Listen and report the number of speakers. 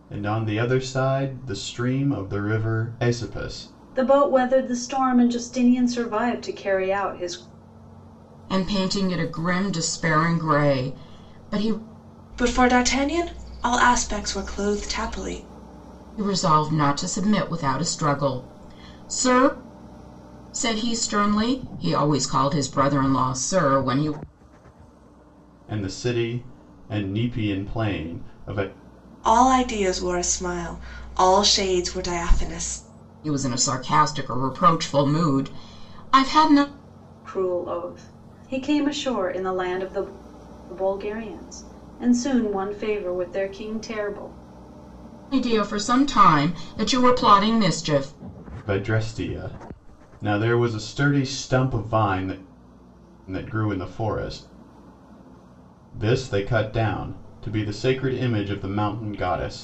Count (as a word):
four